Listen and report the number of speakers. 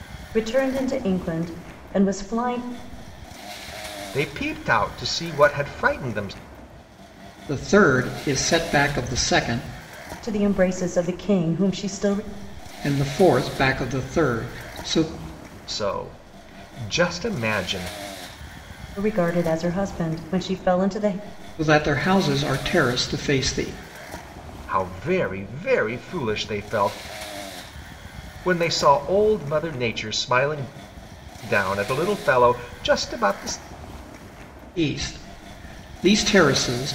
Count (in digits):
3